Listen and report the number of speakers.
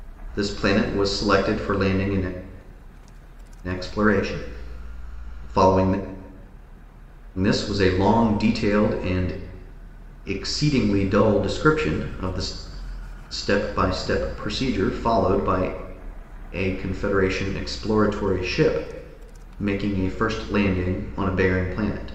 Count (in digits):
1